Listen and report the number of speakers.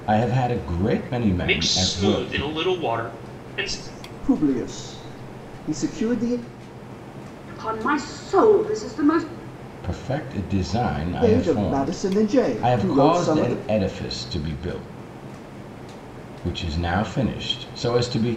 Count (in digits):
4